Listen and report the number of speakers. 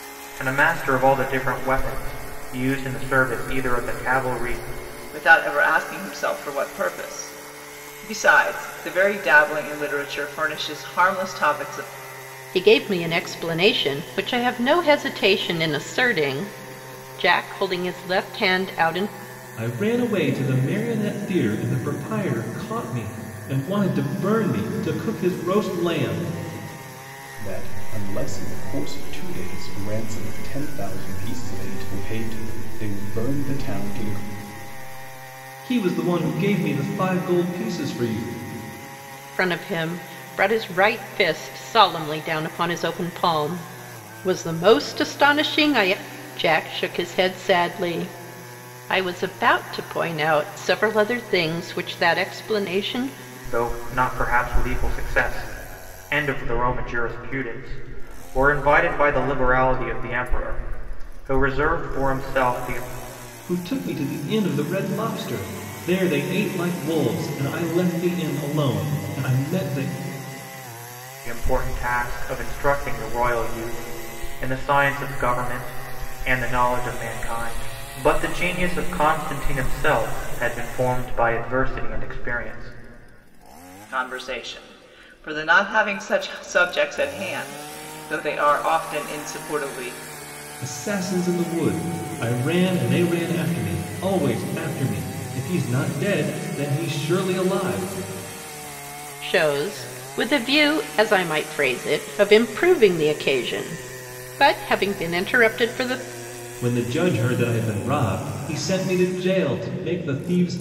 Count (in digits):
5